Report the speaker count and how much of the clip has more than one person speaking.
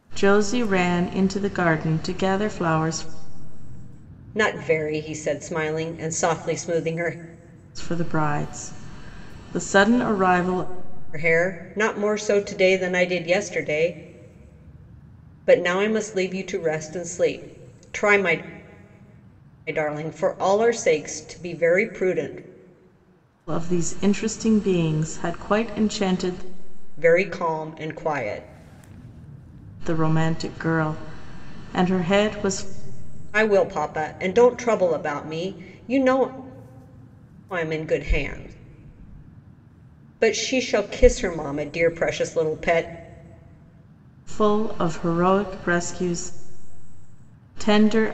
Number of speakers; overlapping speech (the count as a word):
two, no overlap